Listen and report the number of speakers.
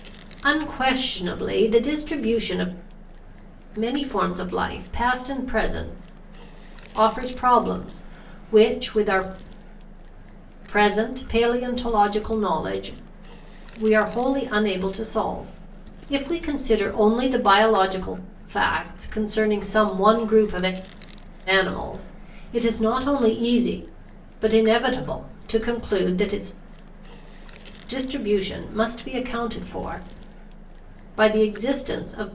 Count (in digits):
1